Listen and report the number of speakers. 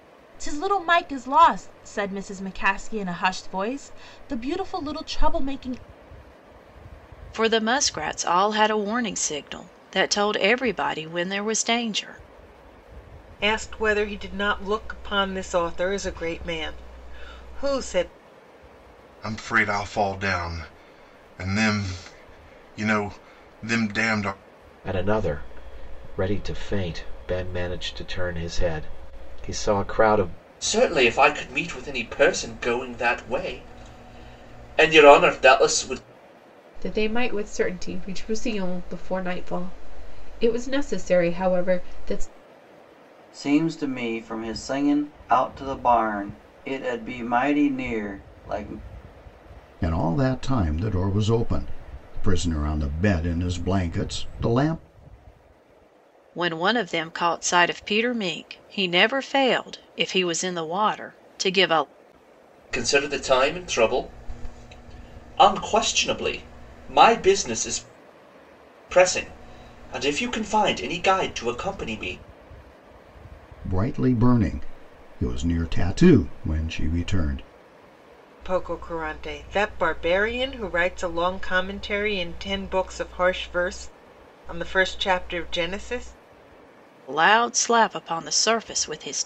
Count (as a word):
nine